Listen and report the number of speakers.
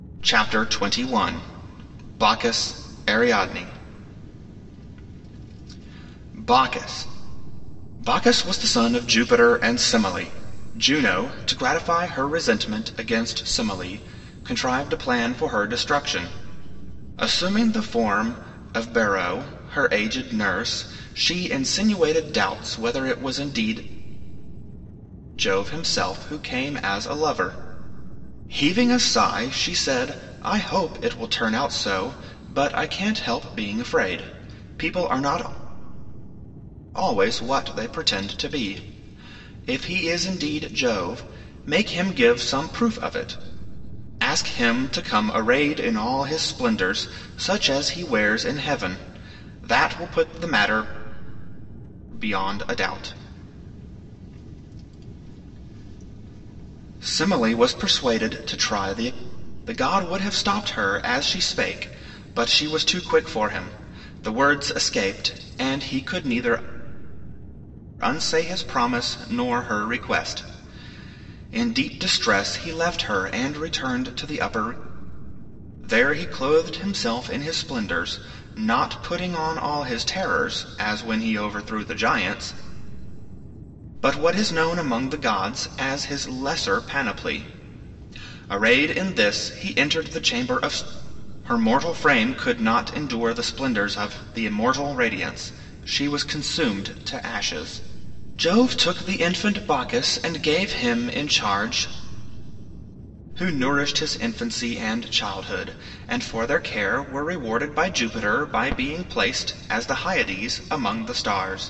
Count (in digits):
1